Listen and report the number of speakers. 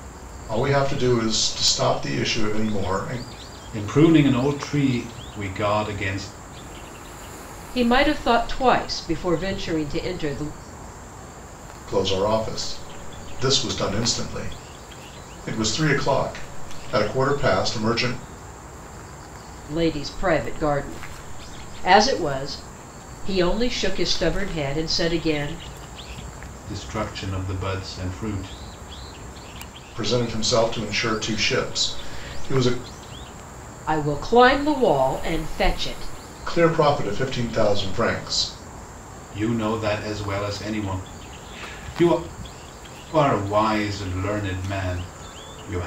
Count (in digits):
3